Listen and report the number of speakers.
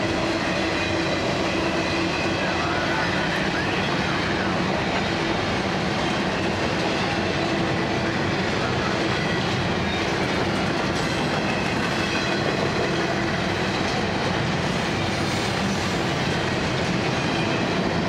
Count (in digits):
0